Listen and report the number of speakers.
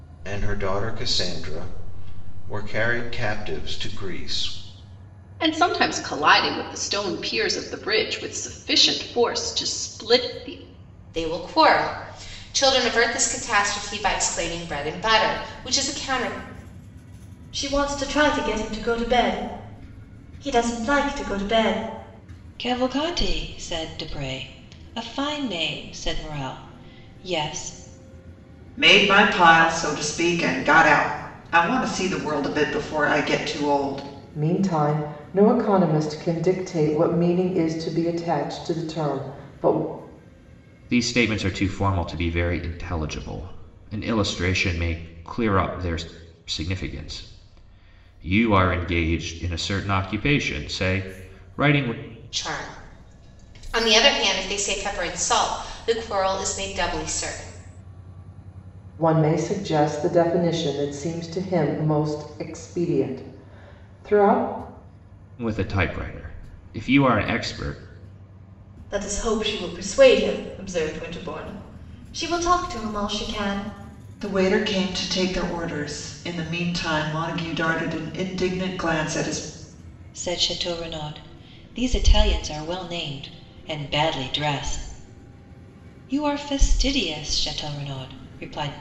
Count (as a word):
eight